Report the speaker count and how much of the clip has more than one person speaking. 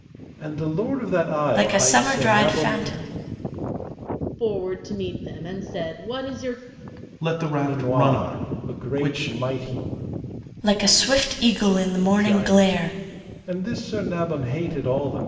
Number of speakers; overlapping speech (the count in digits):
4, about 25%